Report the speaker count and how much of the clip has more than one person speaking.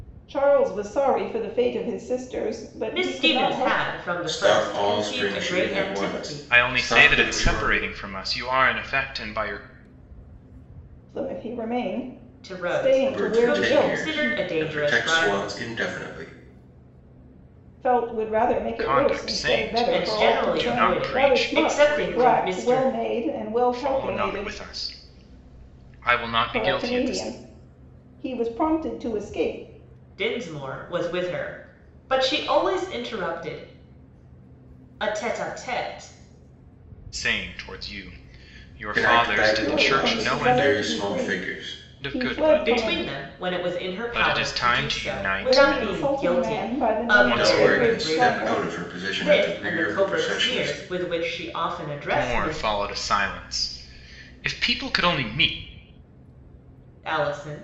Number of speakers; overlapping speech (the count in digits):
4, about 43%